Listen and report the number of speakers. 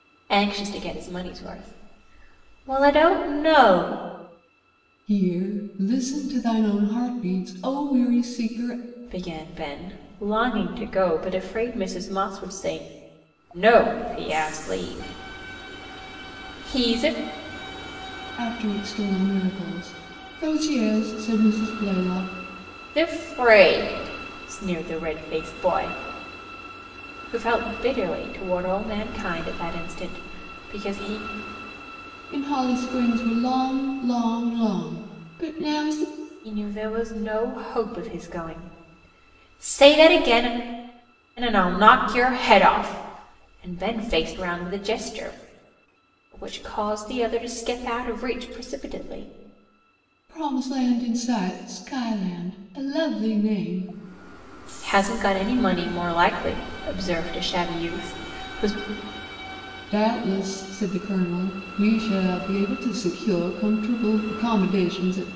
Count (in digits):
2